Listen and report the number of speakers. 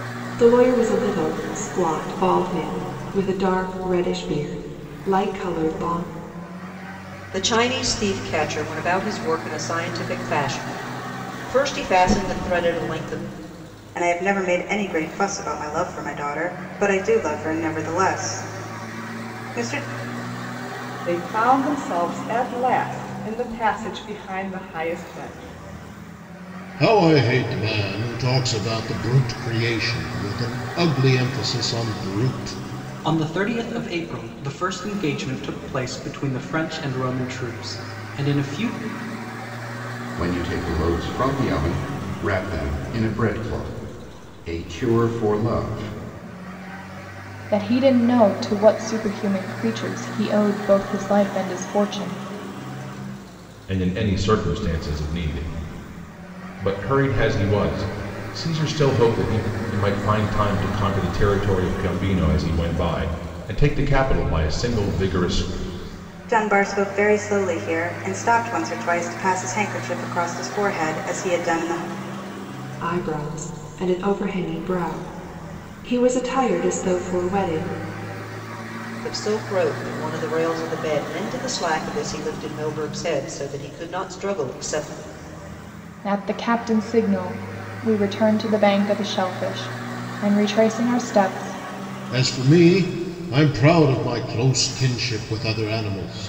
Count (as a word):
nine